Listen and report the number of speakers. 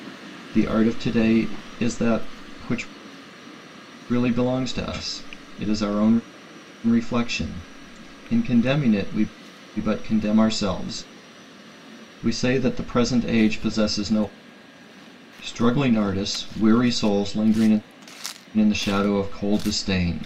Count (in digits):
1